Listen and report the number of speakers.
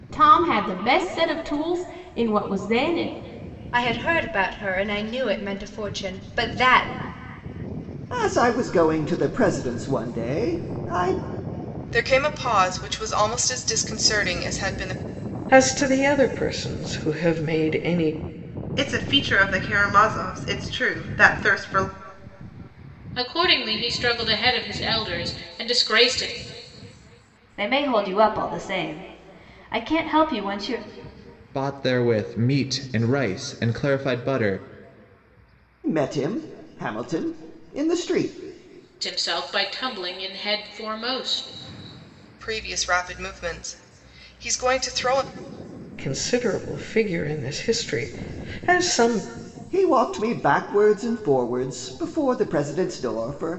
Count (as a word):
nine